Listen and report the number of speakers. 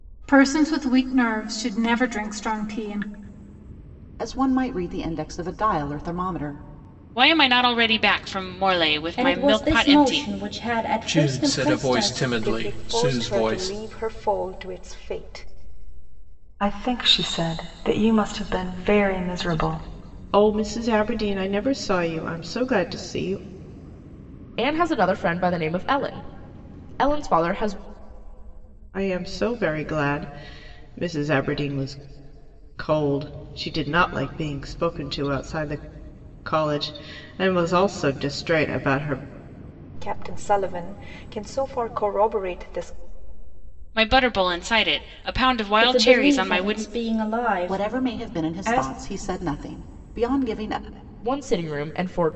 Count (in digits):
9